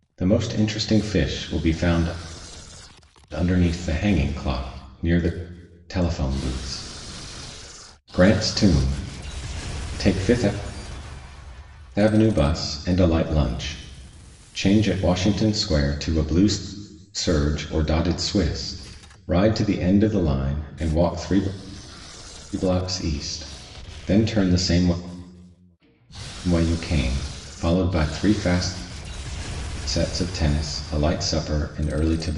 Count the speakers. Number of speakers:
one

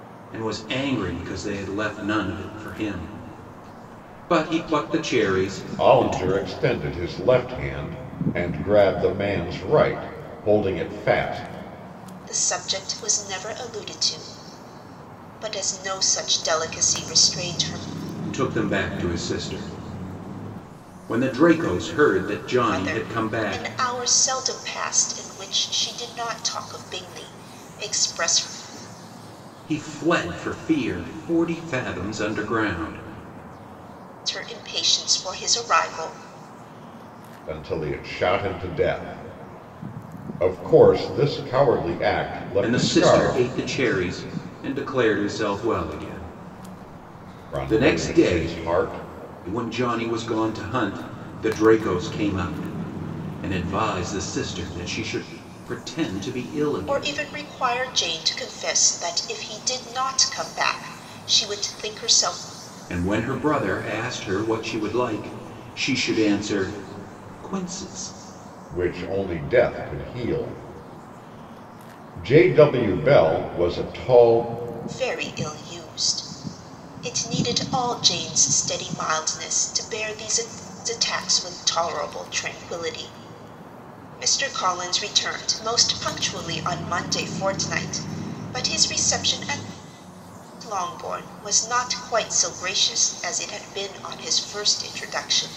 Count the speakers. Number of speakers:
three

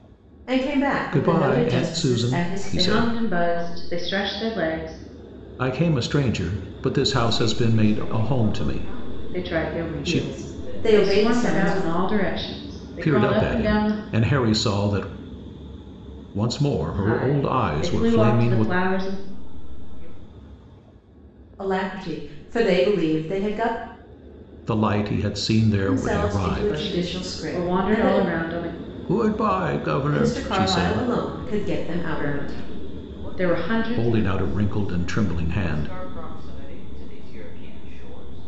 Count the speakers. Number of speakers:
four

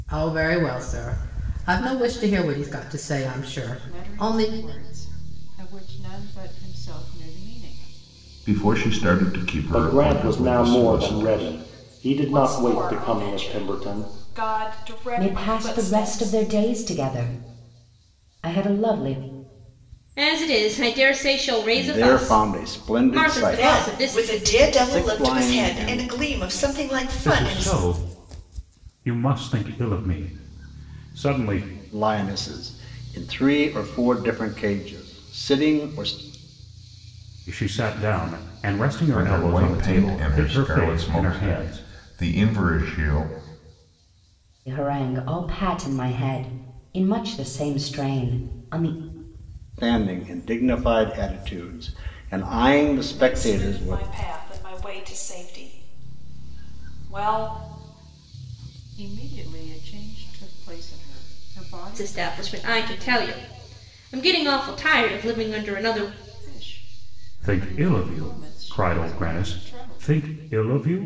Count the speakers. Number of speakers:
ten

